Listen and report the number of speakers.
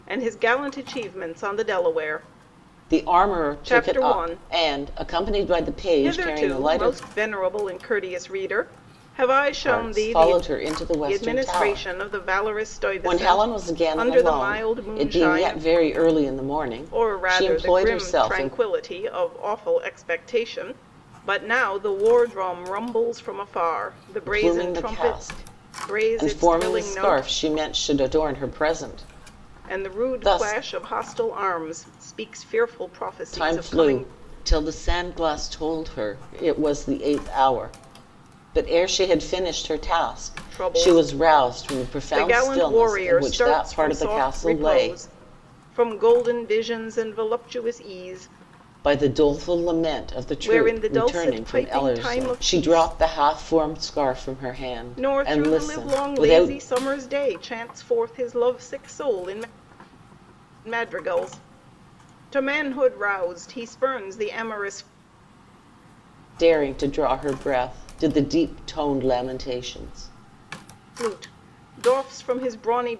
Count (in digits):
2